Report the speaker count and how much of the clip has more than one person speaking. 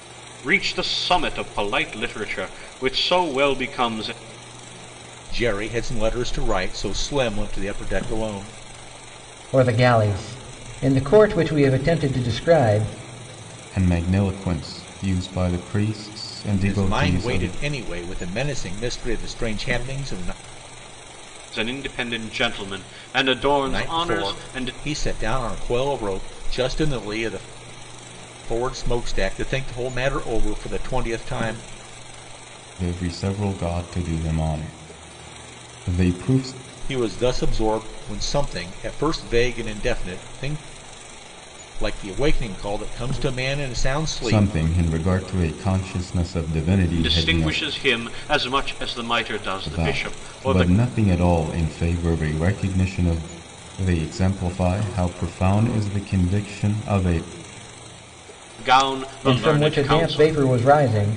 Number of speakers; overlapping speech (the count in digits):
4, about 9%